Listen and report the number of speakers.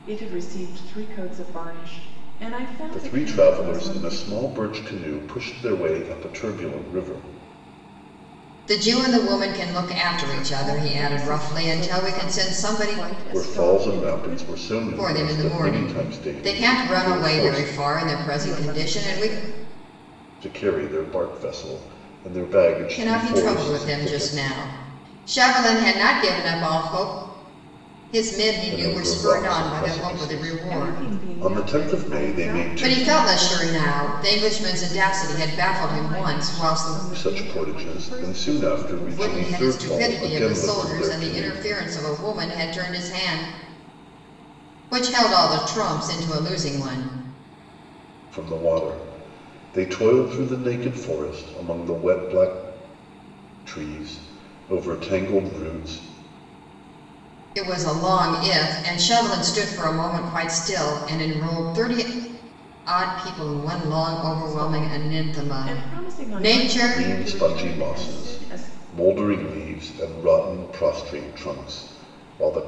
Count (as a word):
three